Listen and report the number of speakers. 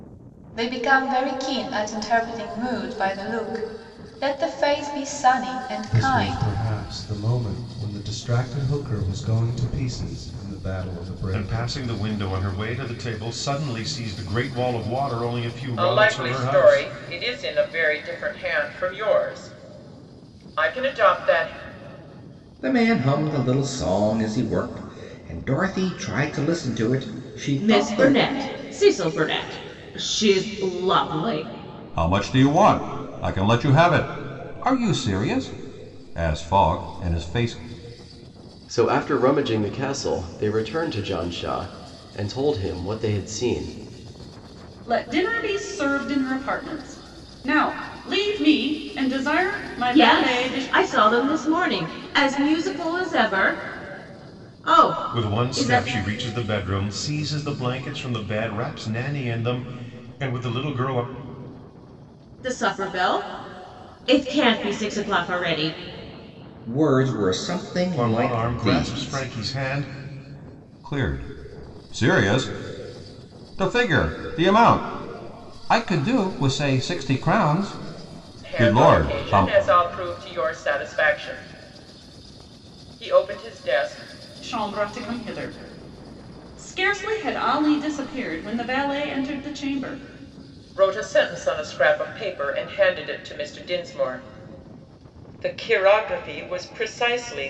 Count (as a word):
nine